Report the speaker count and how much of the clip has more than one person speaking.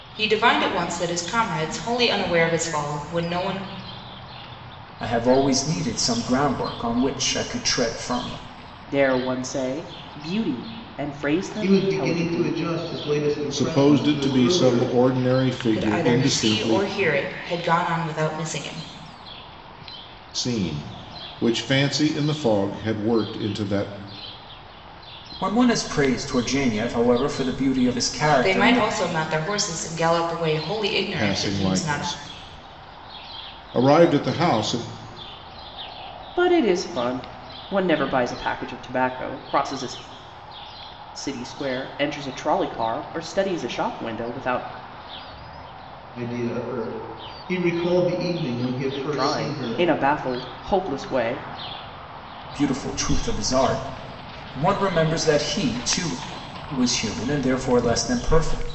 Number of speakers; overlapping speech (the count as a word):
five, about 10%